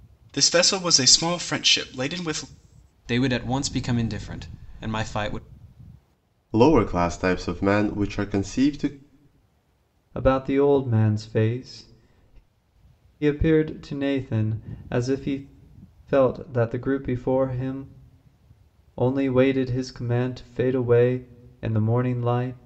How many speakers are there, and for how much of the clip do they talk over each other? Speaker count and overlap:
four, no overlap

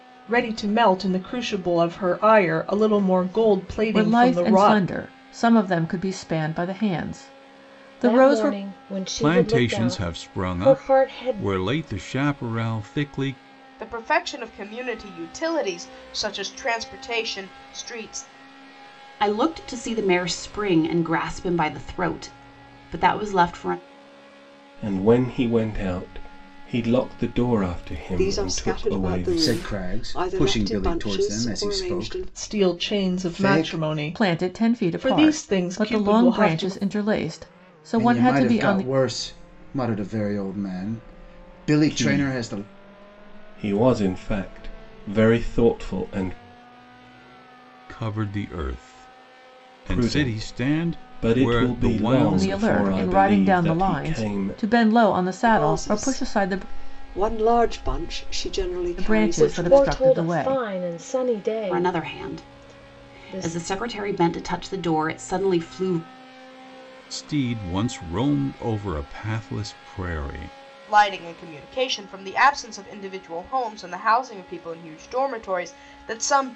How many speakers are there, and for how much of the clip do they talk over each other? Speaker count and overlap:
nine, about 31%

